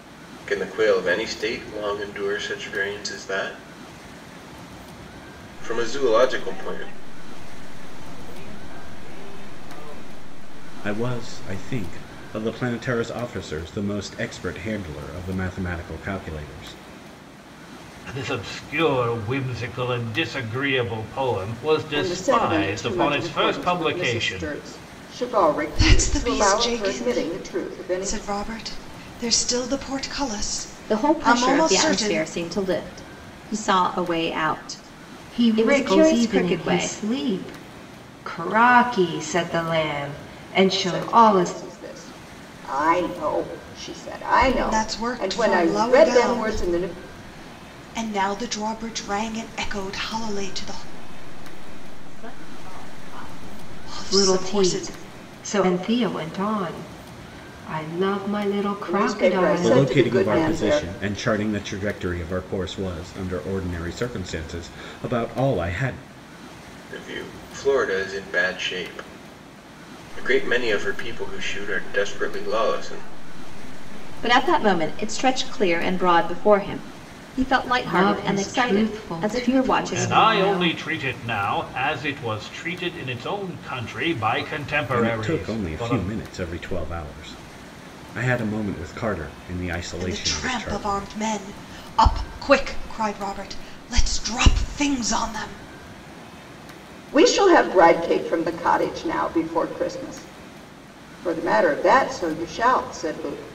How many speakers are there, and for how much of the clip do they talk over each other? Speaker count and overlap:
8, about 27%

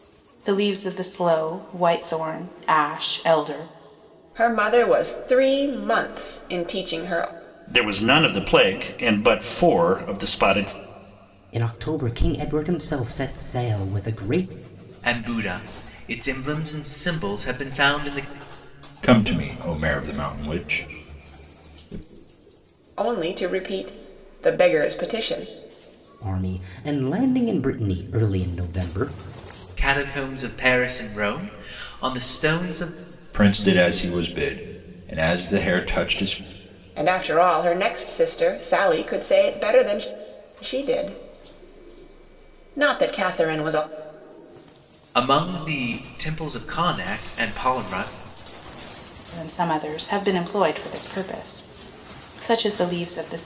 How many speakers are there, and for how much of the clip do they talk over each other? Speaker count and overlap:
6, no overlap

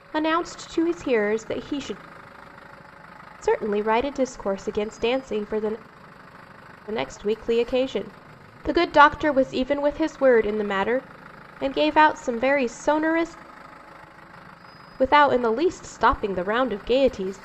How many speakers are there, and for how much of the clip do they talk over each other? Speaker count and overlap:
1, no overlap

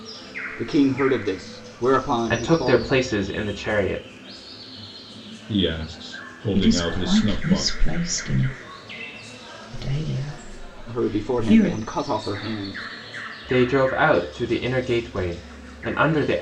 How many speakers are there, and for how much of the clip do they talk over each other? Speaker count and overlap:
4, about 18%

